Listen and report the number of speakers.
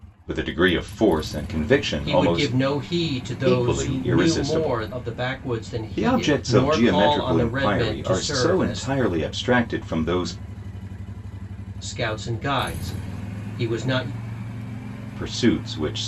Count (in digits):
2